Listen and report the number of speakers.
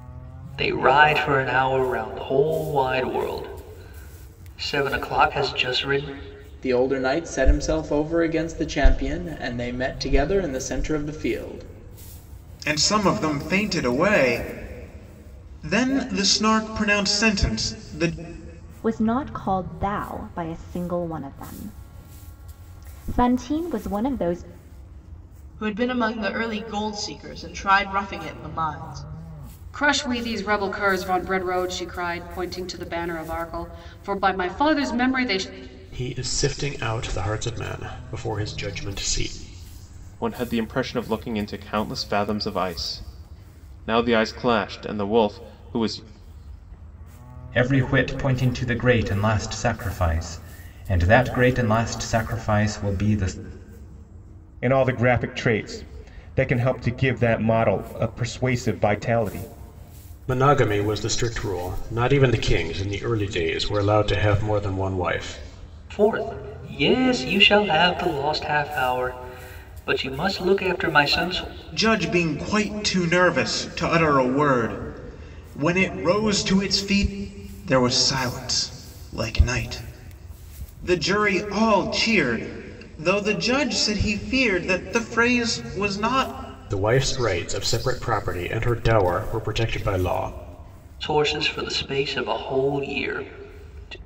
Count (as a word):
ten